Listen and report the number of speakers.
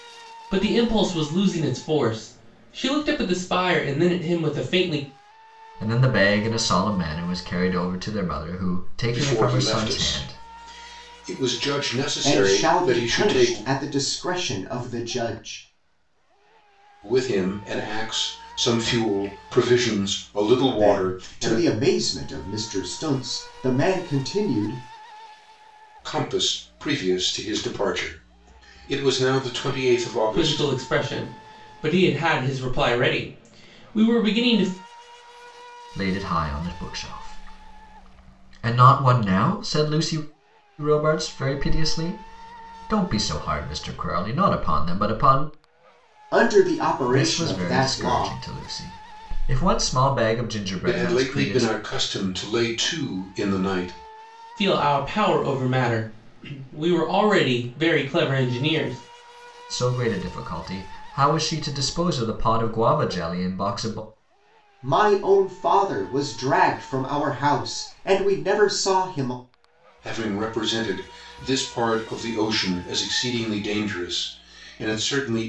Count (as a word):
four